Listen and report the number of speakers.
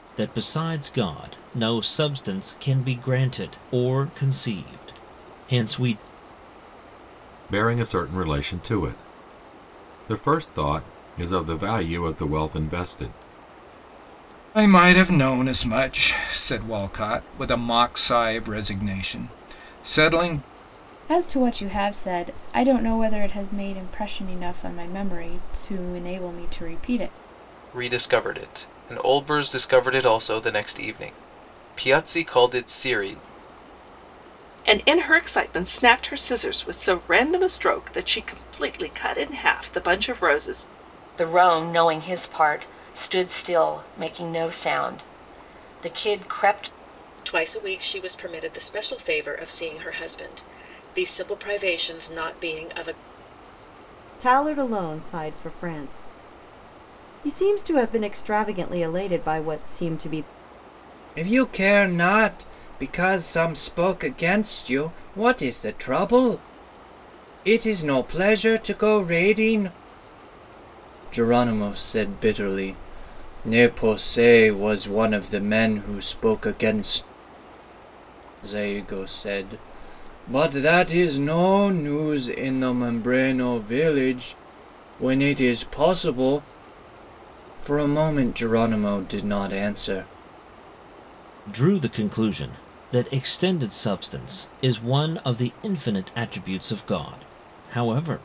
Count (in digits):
10